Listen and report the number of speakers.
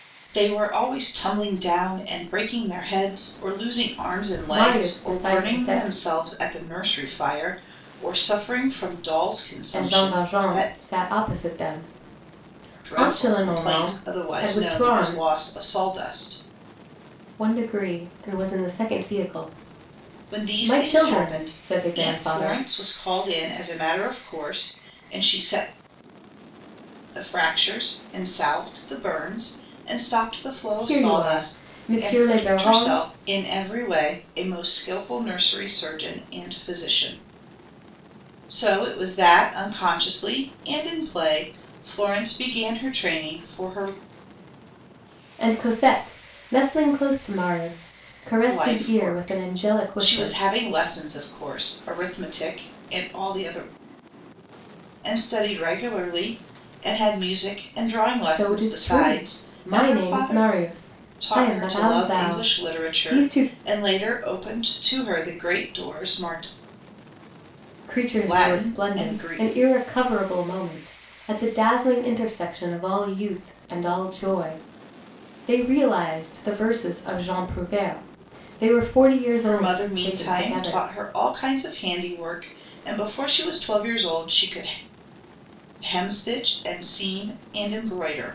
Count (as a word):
two